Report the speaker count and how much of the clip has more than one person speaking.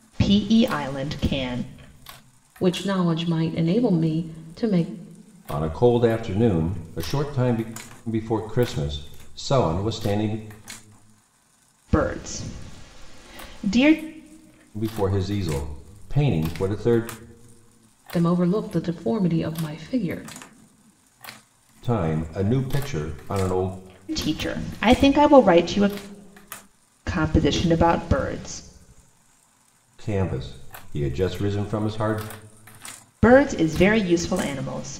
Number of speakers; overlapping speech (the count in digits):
3, no overlap